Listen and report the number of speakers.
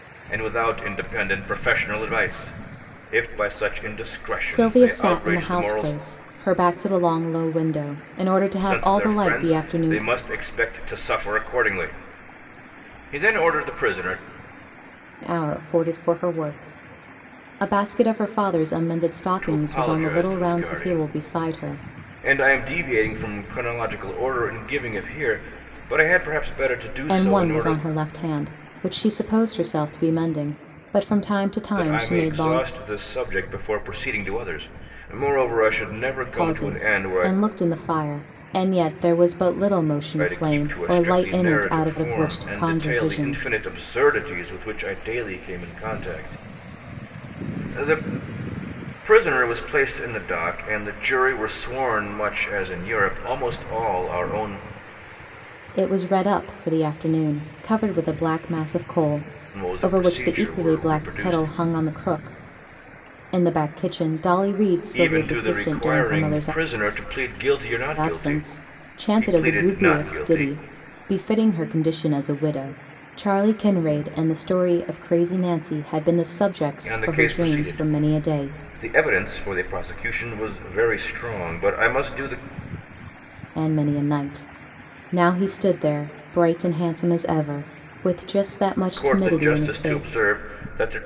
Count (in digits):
2